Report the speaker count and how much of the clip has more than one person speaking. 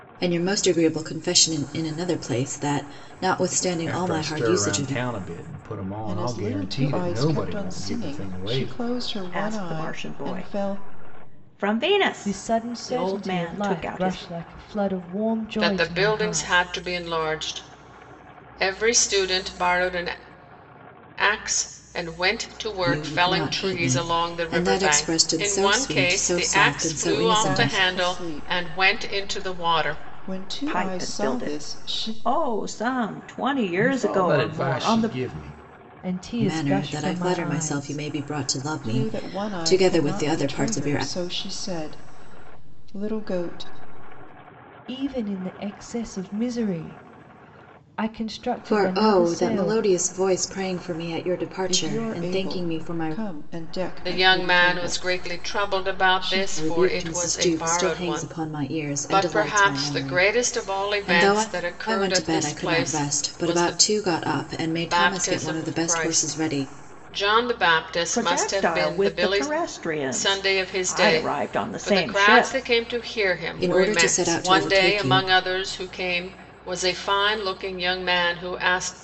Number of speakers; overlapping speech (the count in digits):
6, about 52%